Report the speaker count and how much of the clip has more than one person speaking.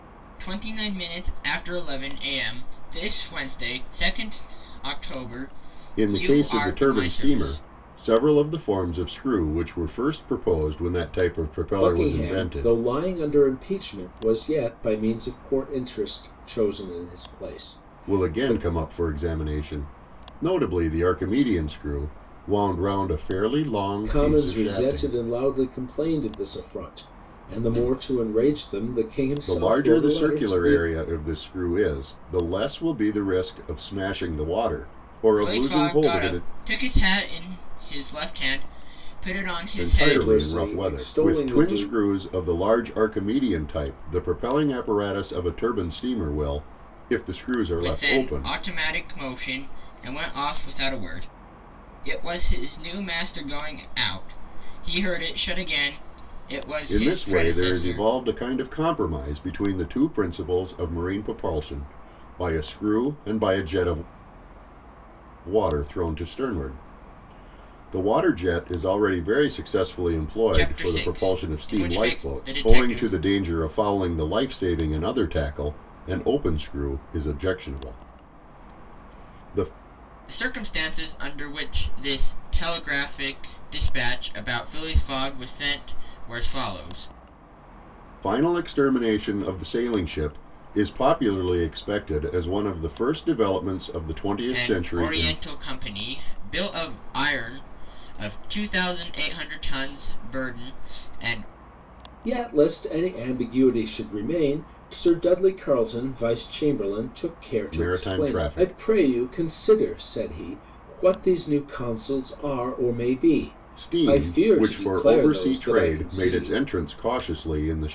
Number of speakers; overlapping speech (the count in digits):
3, about 16%